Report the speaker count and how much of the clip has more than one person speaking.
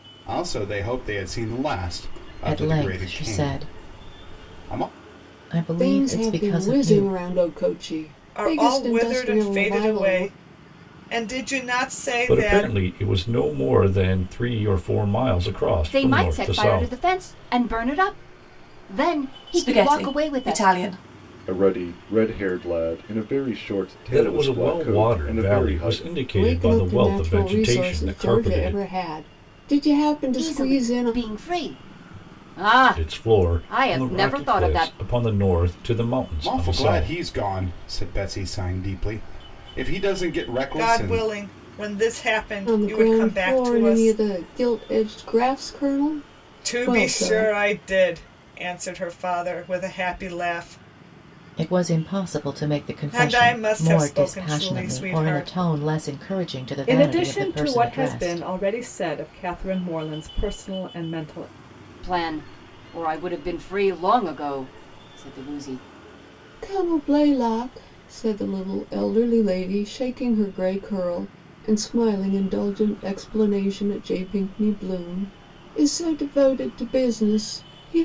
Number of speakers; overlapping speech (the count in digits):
8, about 31%